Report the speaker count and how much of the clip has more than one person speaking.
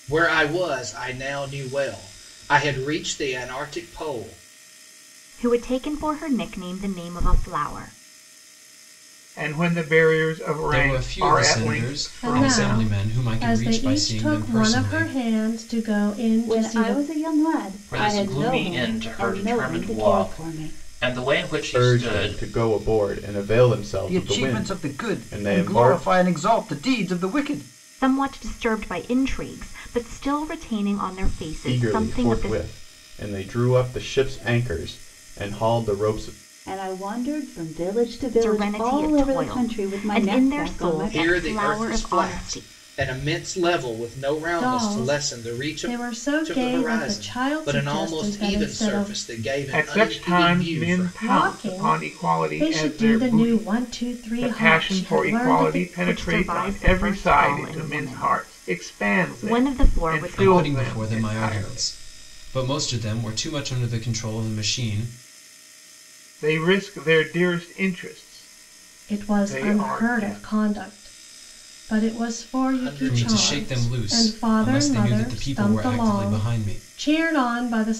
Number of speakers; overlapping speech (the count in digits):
9, about 48%